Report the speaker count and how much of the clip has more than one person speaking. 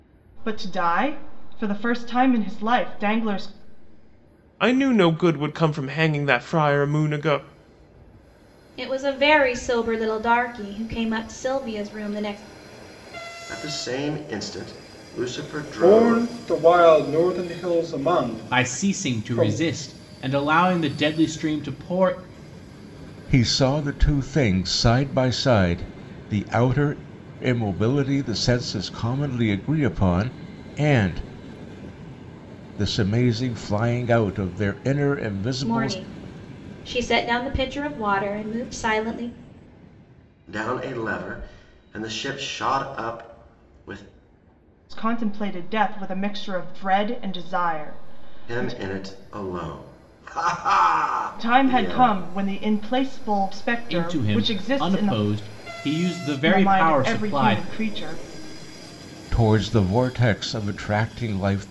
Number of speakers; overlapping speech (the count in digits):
7, about 9%